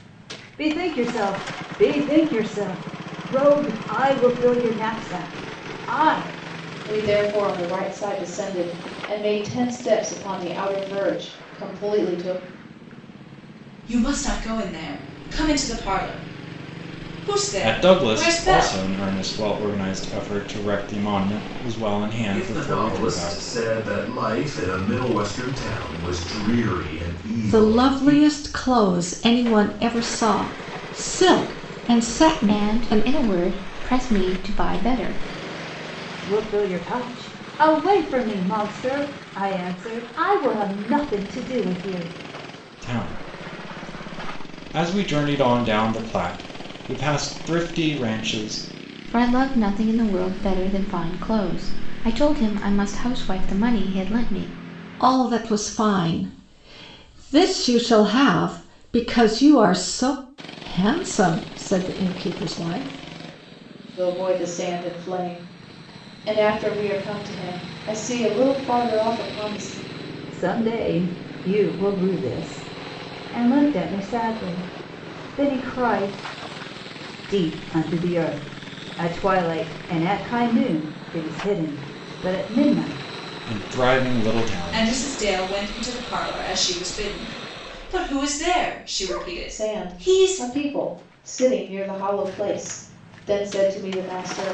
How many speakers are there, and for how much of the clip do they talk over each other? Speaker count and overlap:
seven, about 5%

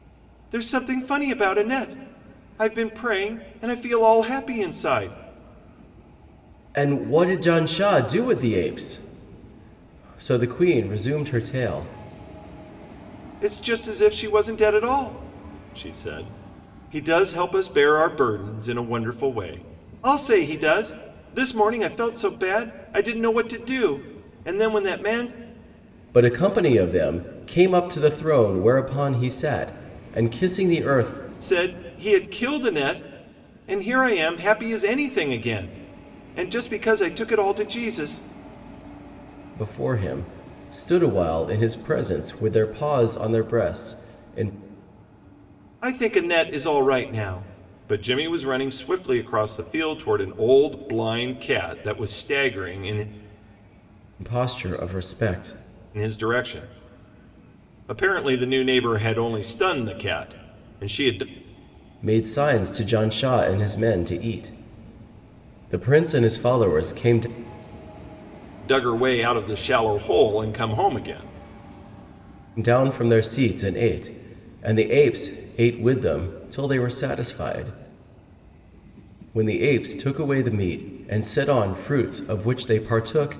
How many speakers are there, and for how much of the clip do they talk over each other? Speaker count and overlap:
two, no overlap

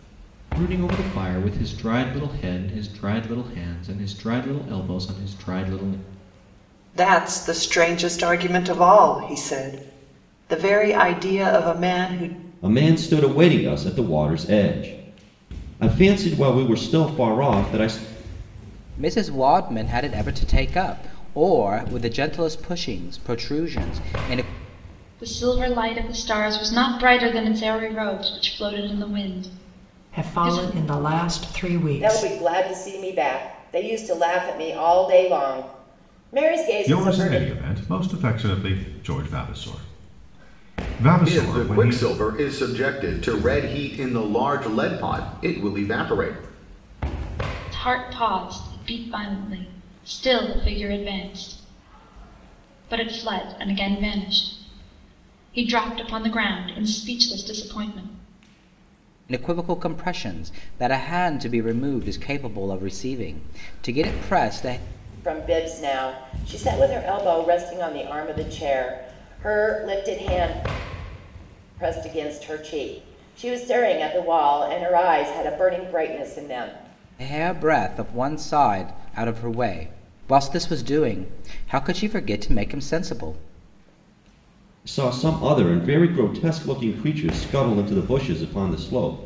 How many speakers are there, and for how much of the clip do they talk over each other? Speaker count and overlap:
nine, about 3%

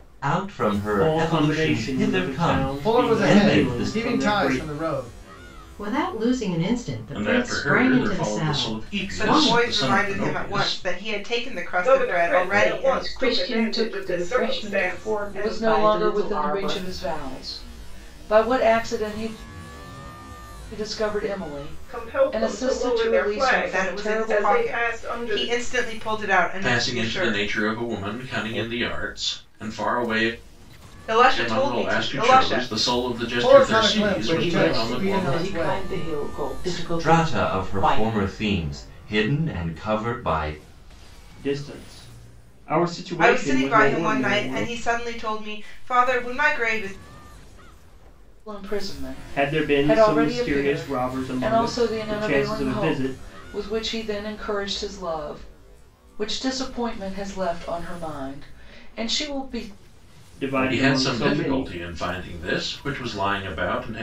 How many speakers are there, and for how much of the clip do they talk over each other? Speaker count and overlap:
nine, about 45%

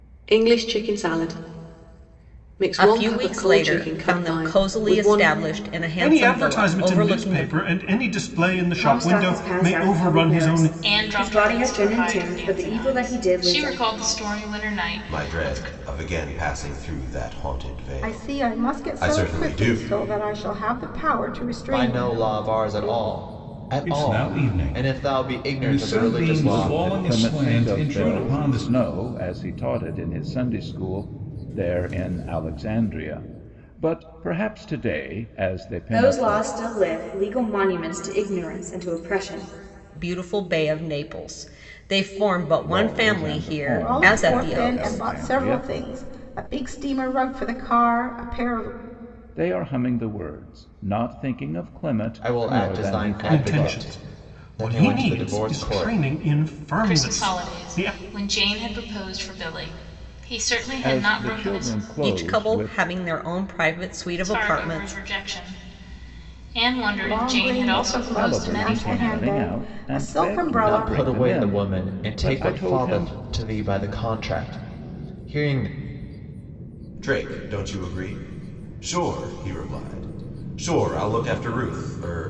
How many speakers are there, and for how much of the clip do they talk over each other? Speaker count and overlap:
ten, about 43%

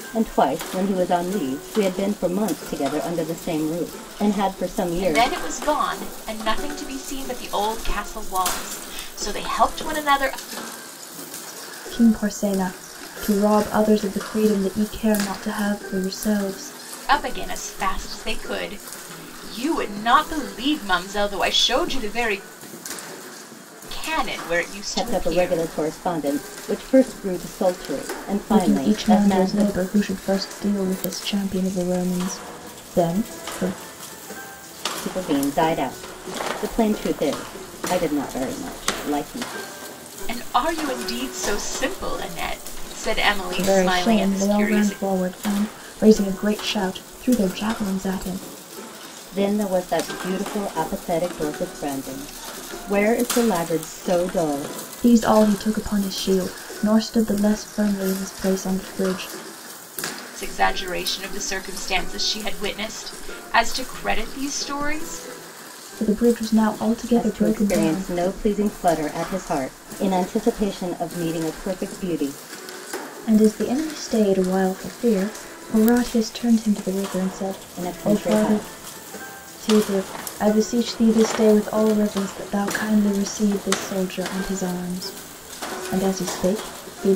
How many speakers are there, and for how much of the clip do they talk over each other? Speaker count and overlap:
three, about 7%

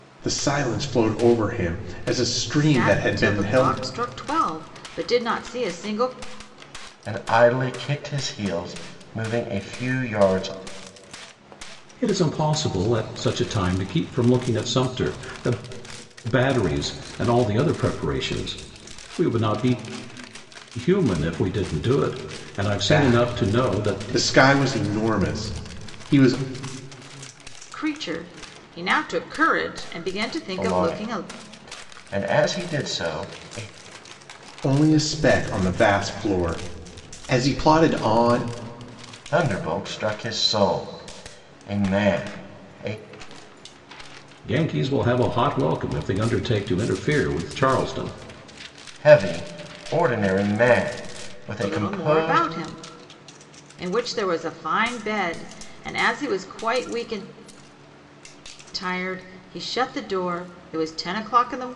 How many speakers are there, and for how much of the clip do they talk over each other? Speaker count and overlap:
four, about 7%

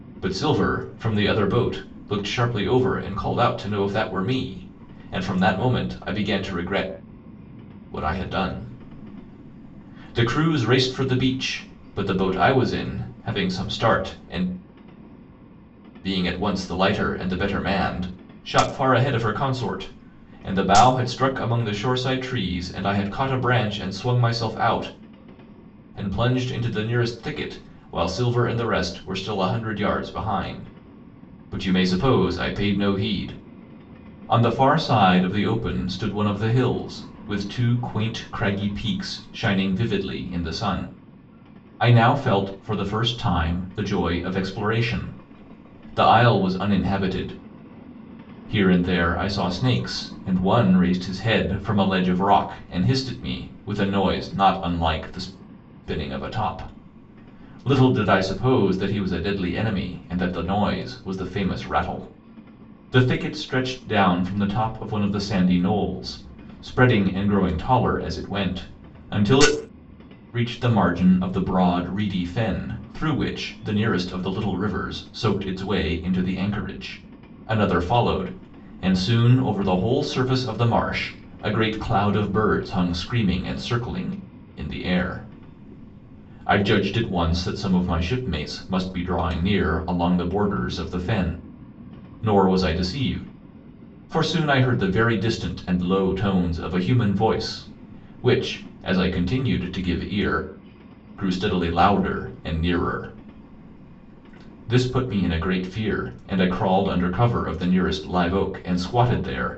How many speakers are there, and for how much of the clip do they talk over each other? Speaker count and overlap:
one, no overlap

